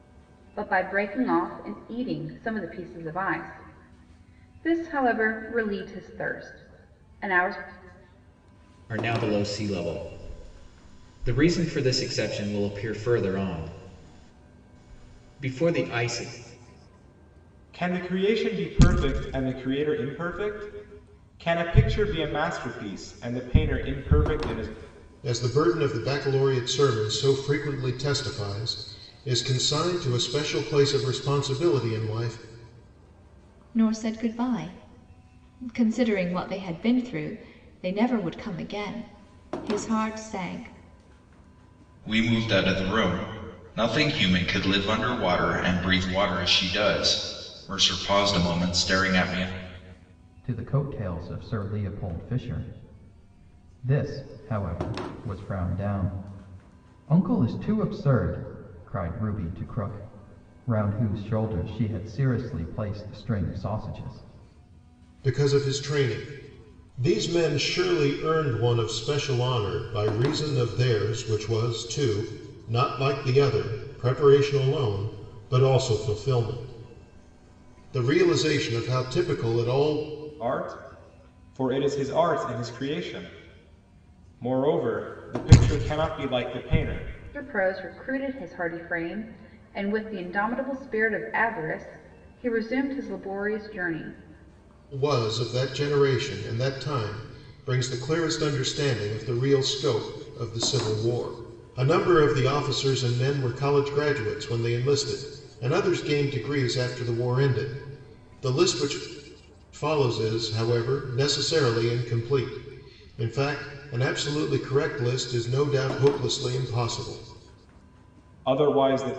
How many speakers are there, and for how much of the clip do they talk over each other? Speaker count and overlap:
7, no overlap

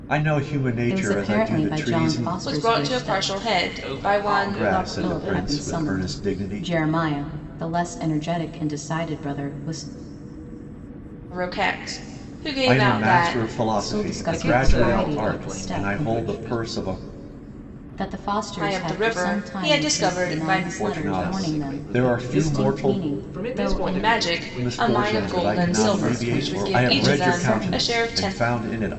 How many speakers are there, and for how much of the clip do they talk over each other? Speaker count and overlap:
4, about 65%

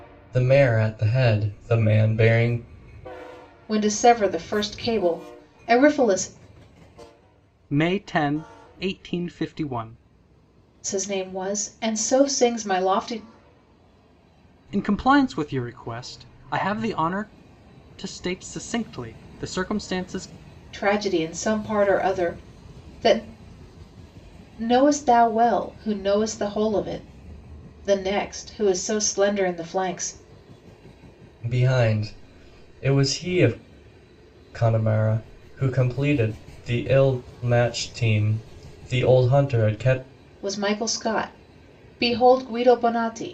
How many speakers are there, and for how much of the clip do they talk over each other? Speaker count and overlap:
3, no overlap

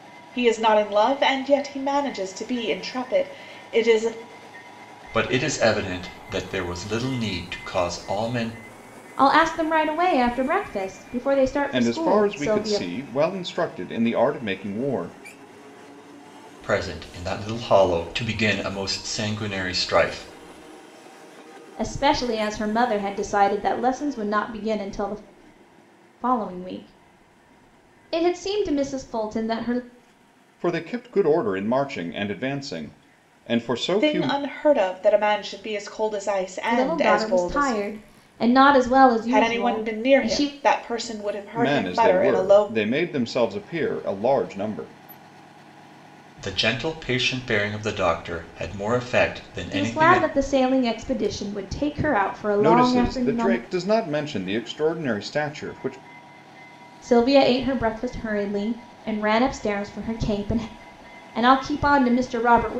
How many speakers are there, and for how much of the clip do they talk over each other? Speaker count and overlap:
4, about 11%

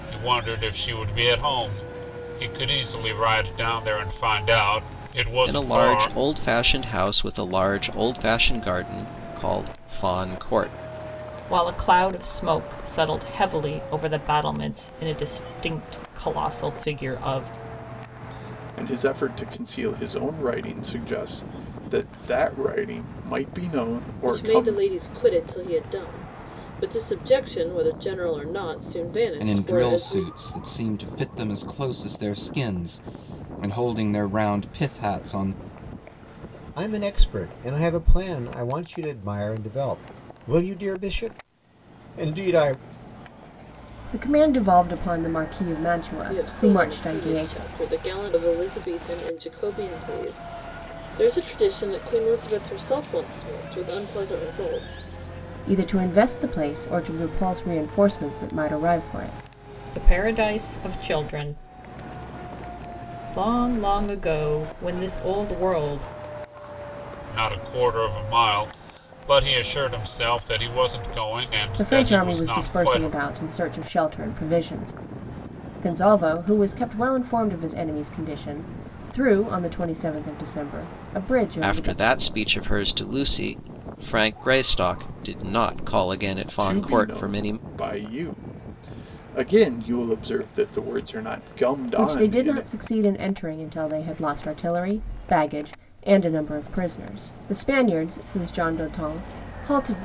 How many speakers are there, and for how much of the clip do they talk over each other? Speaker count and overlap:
8, about 7%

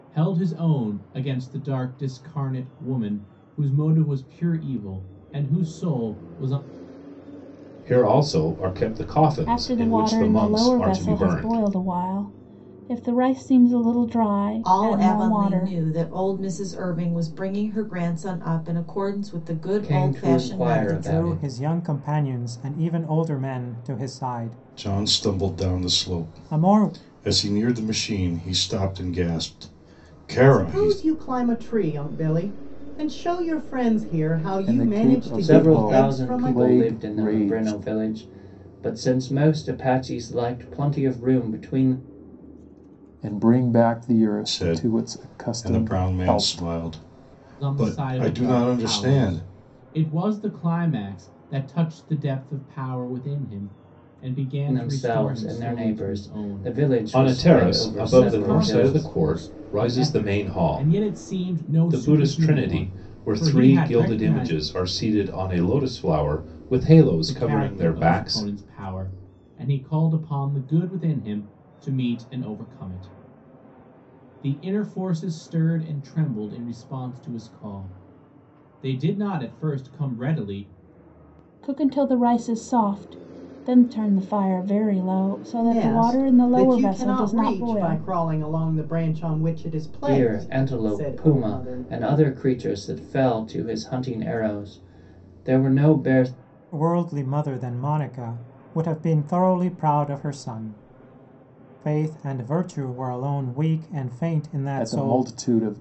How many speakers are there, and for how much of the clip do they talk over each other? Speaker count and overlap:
9, about 28%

